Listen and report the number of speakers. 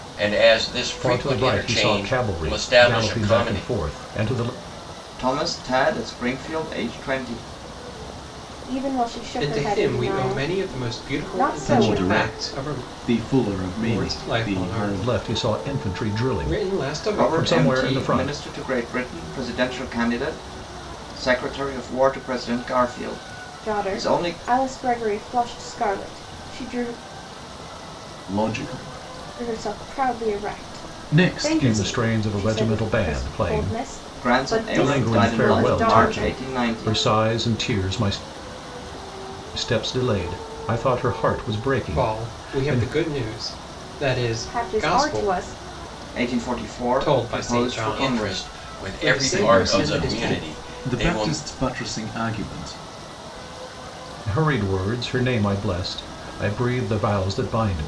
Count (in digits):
6